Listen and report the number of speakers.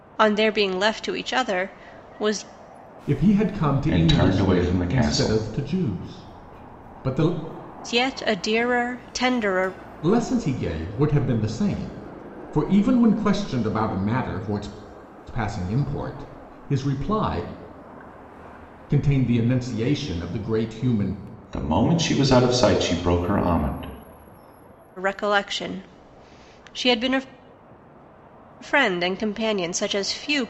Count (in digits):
3